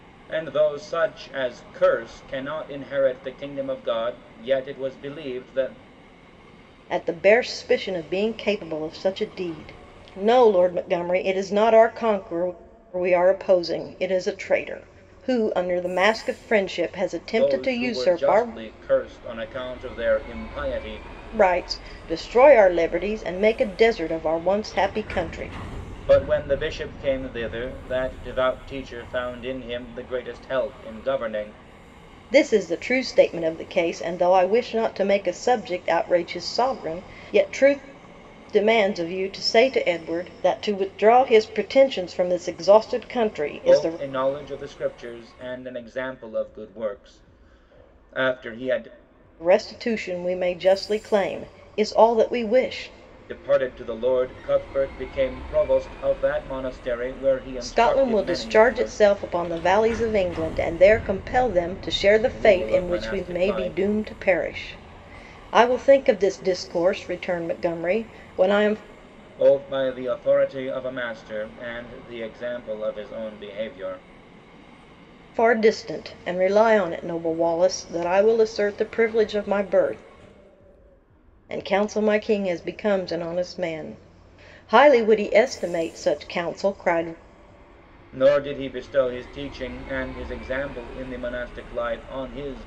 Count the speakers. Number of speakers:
two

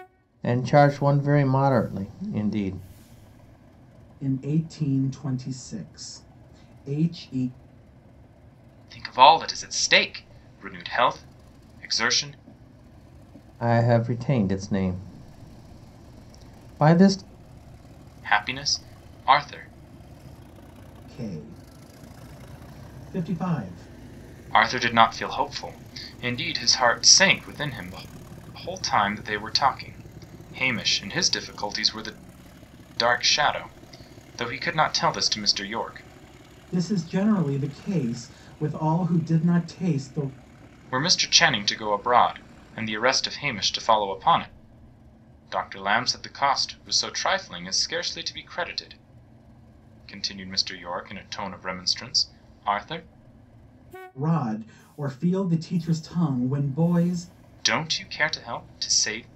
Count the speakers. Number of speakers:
three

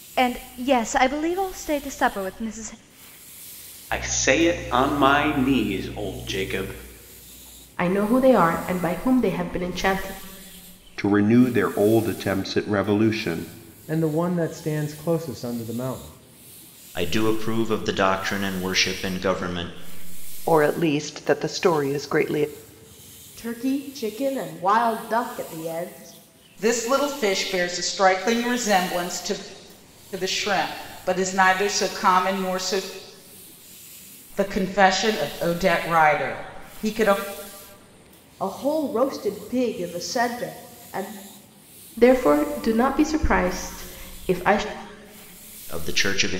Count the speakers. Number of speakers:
nine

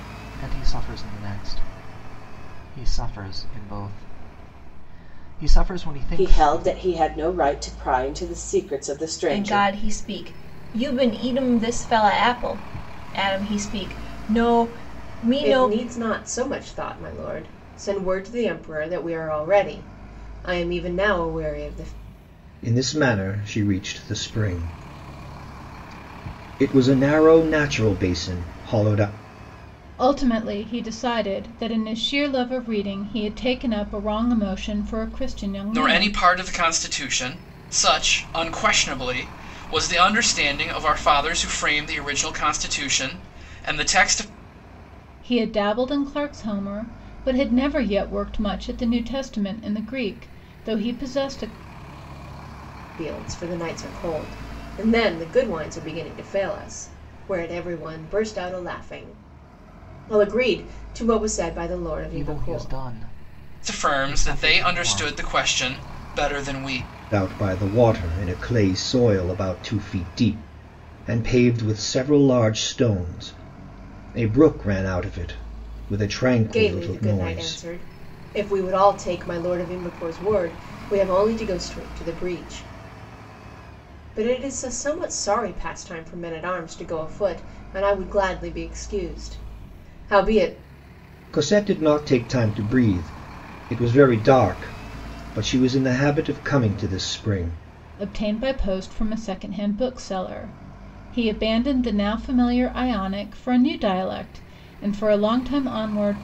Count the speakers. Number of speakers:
seven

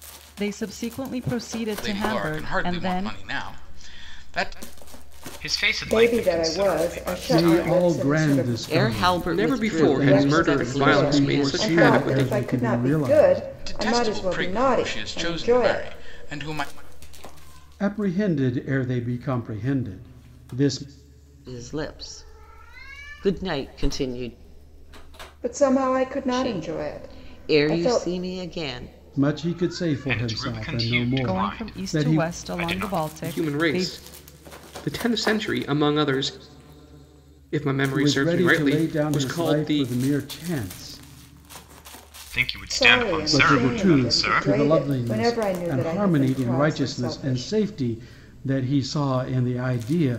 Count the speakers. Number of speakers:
seven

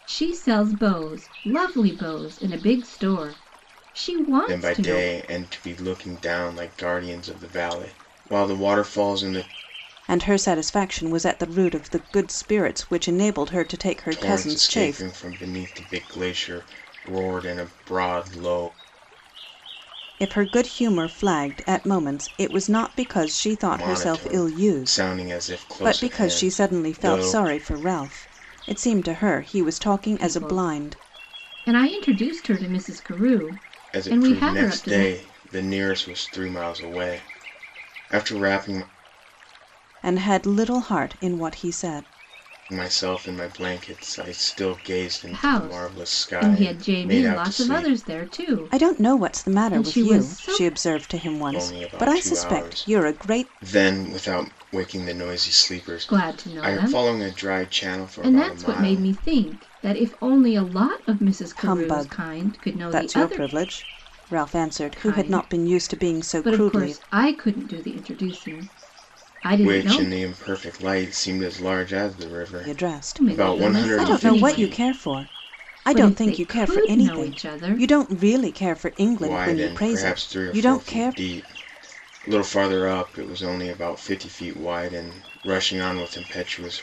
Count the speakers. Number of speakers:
three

